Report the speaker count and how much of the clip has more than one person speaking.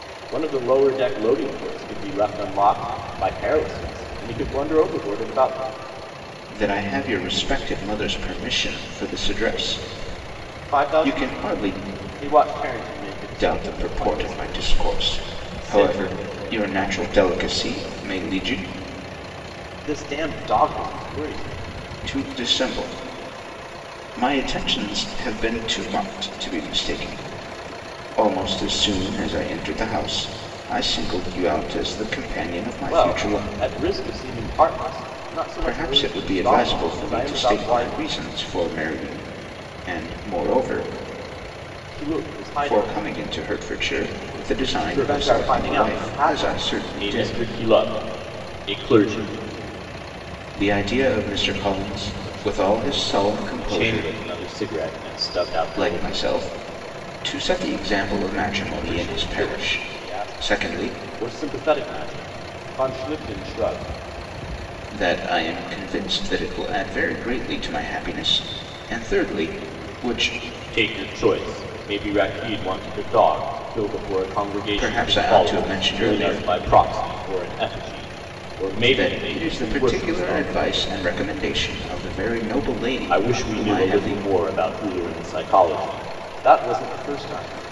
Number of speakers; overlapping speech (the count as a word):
two, about 22%